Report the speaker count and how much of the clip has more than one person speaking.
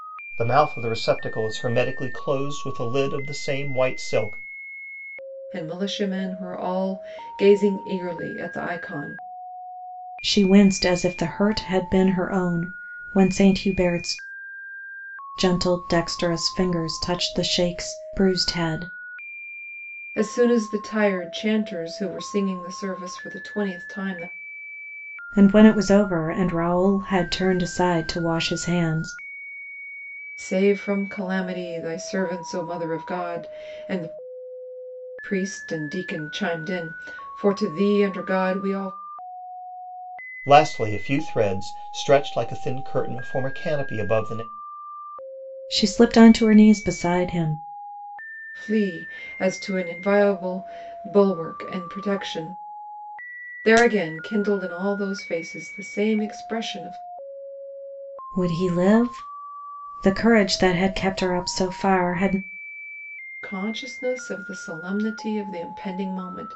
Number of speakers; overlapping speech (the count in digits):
3, no overlap